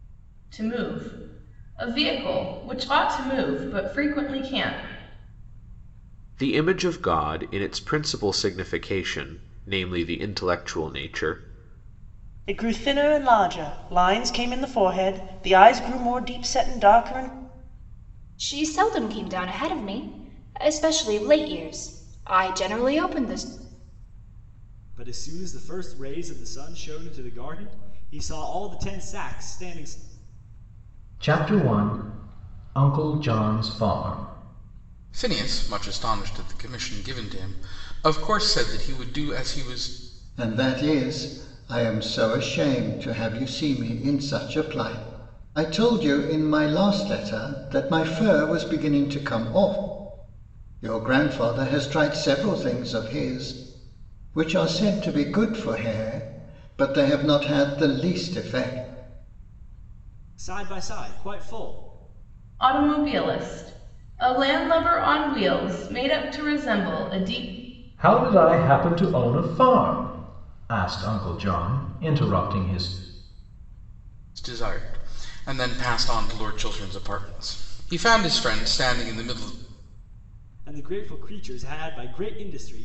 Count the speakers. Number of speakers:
eight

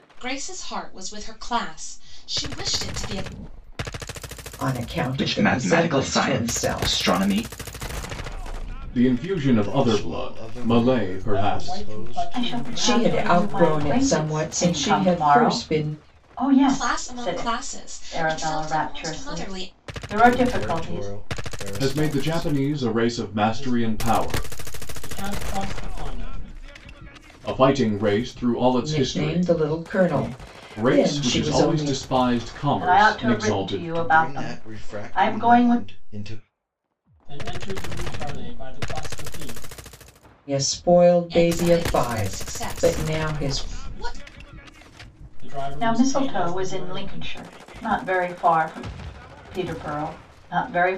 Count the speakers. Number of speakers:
seven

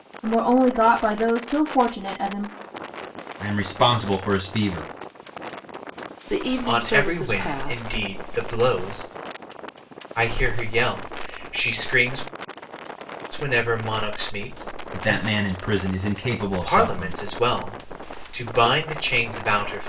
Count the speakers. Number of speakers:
four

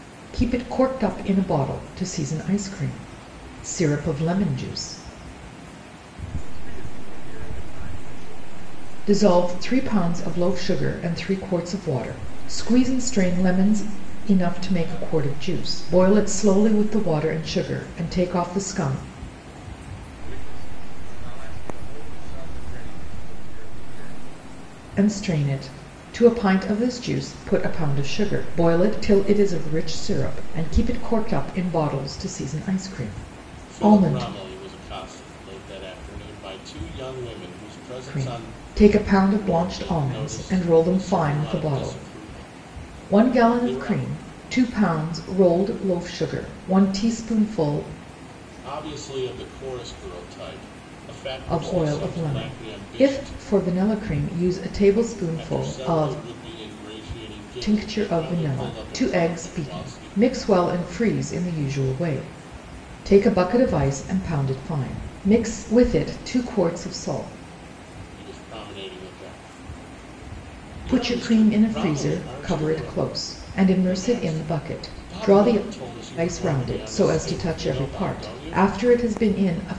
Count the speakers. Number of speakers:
two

